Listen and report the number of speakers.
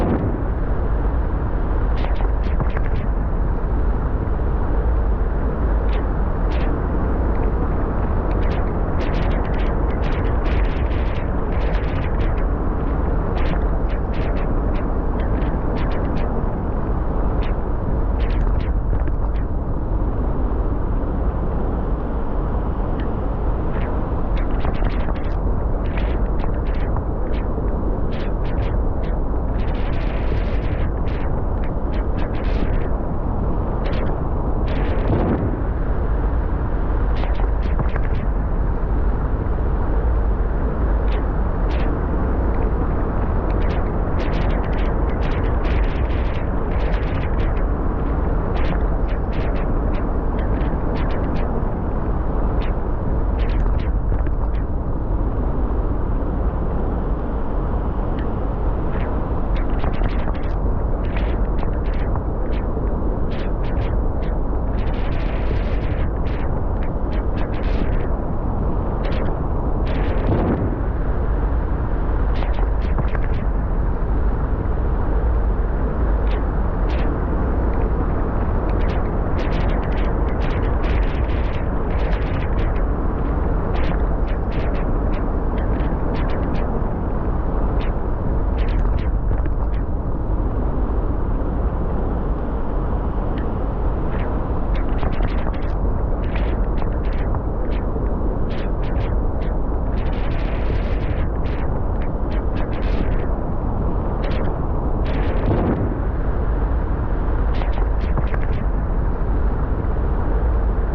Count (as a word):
zero